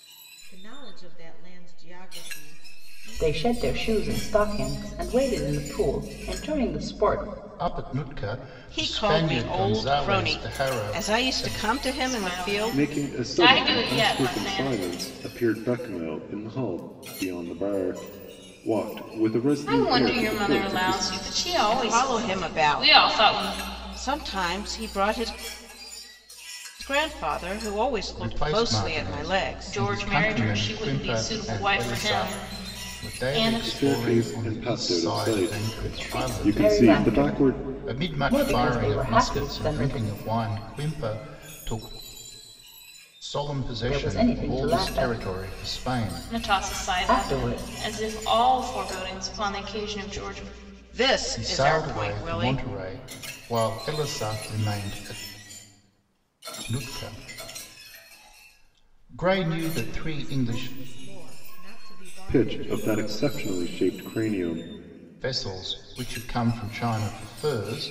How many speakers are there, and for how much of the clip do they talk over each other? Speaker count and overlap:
six, about 43%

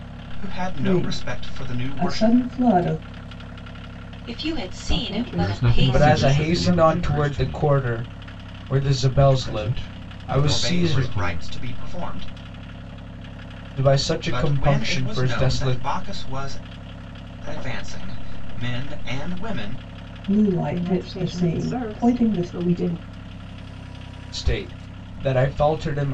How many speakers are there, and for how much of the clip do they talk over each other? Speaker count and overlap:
six, about 40%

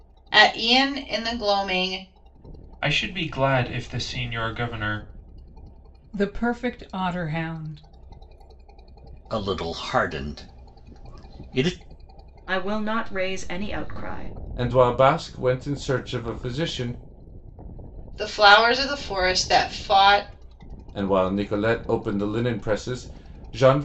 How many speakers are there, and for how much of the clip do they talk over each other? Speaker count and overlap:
six, no overlap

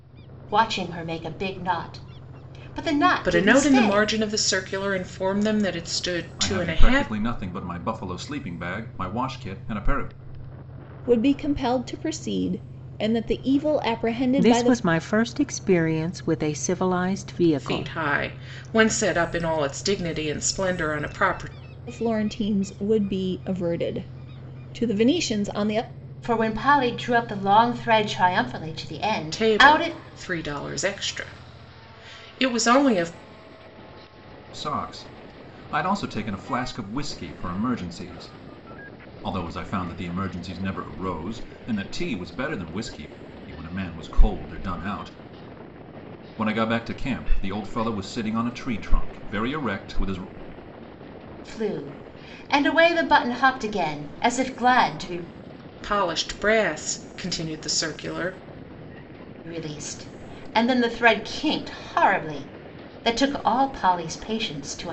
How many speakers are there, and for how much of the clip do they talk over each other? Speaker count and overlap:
five, about 5%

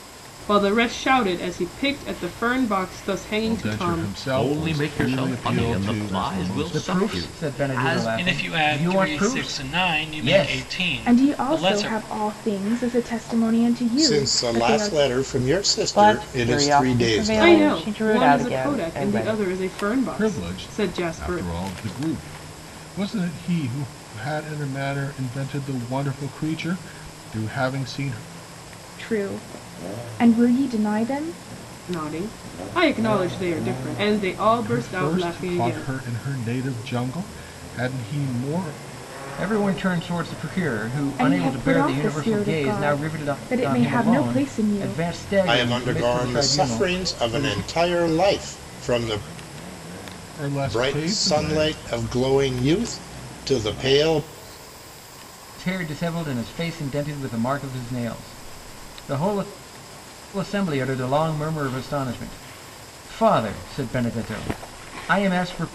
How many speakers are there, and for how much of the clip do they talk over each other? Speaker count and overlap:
eight, about 34%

